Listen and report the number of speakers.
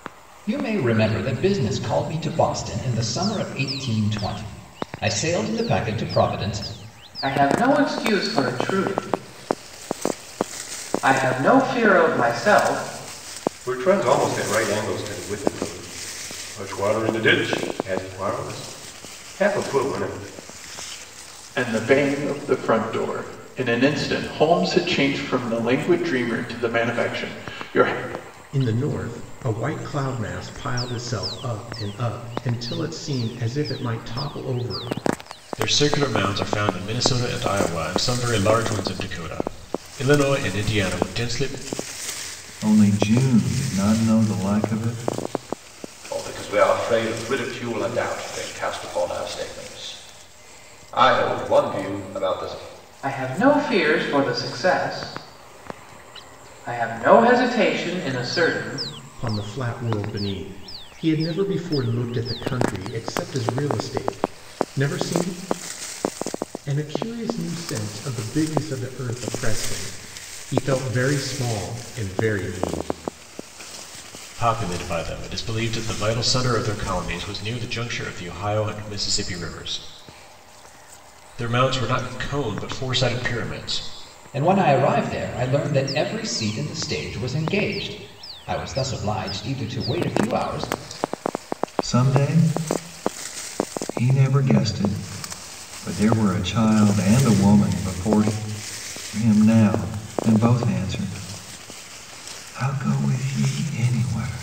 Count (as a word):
eight